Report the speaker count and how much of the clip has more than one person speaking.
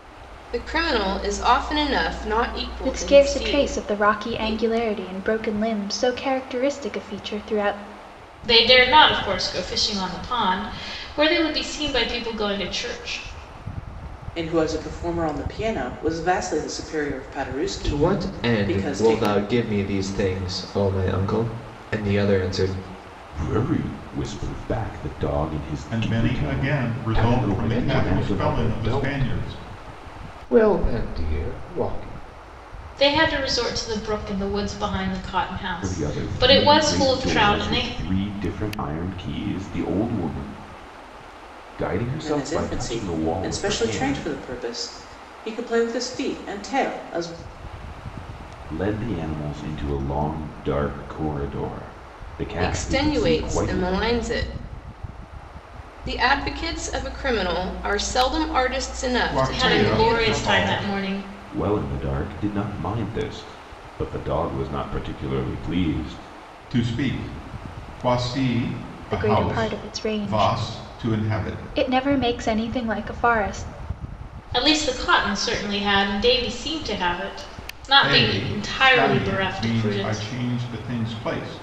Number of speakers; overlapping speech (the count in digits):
8, about 24%